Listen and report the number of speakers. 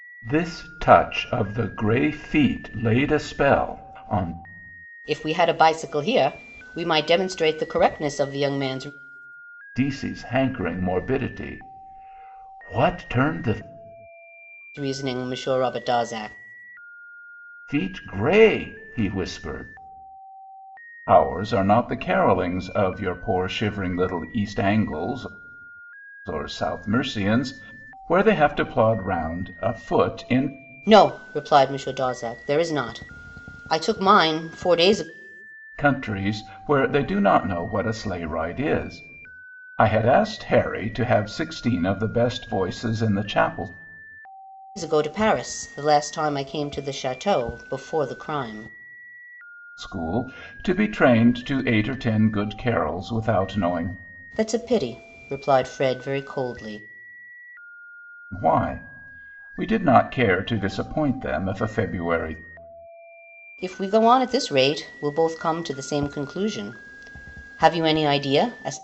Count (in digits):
2